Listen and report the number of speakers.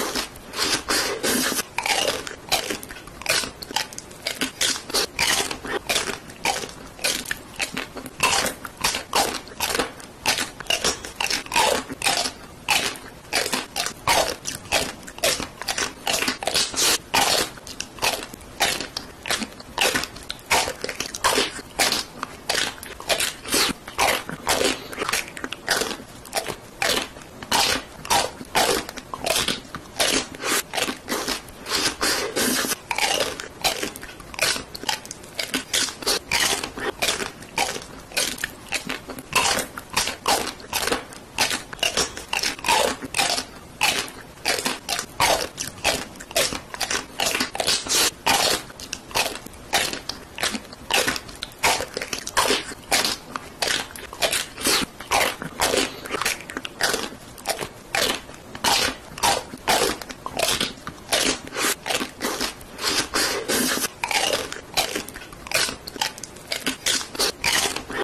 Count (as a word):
zero